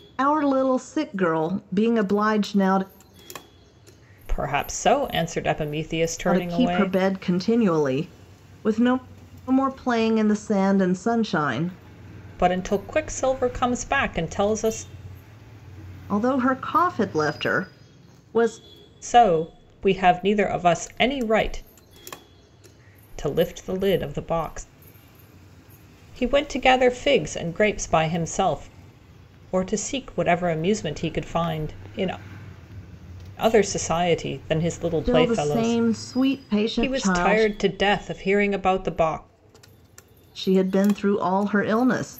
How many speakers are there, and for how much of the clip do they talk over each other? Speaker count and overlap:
2, about 5%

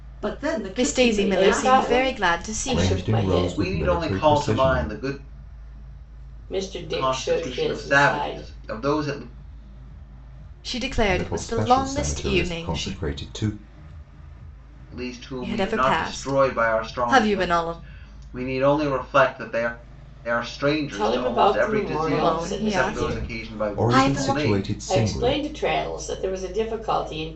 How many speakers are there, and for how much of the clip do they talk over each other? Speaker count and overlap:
5, about 53%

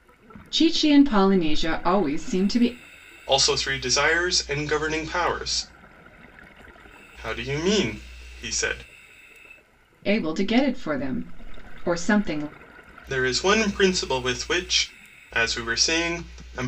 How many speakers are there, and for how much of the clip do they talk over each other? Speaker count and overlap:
2, no overlap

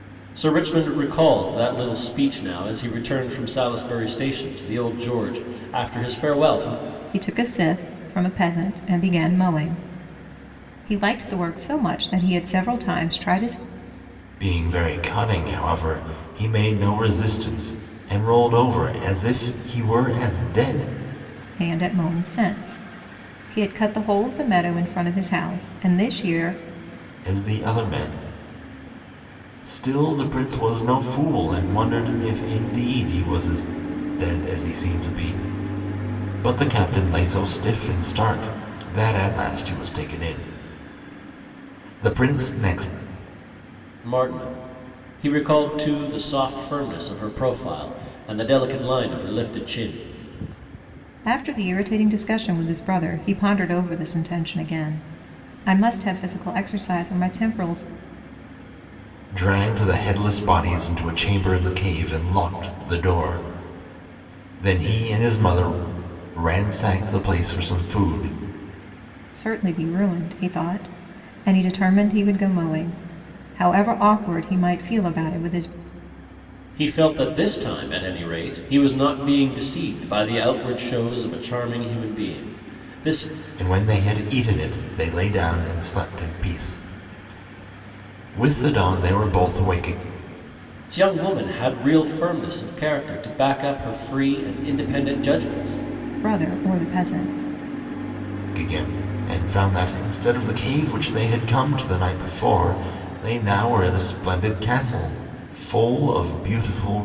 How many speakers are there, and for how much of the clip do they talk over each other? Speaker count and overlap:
3, no overlap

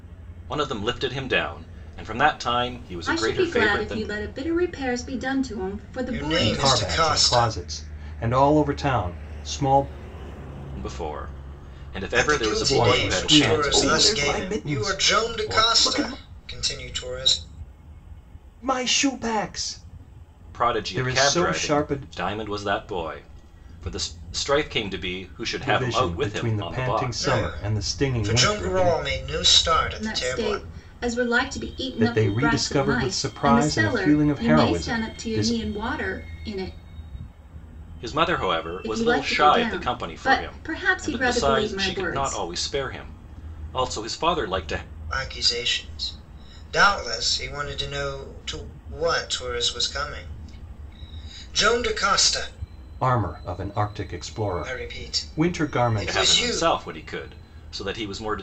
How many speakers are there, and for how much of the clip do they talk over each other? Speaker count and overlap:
4, about 36%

